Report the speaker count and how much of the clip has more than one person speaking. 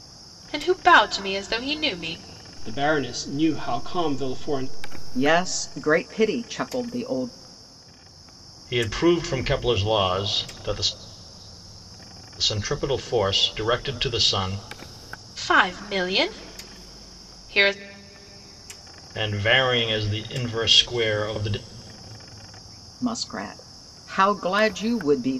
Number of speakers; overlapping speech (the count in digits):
4, no overlap